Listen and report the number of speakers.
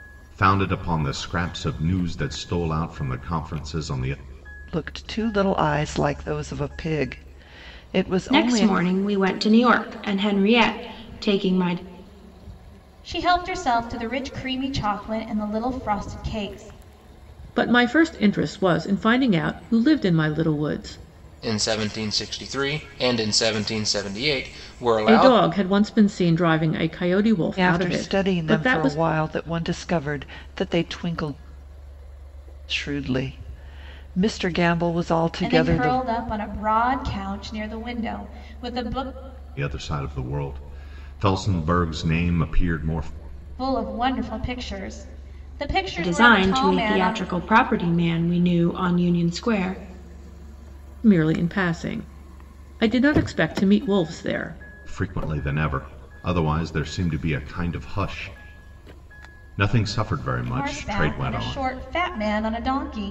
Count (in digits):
6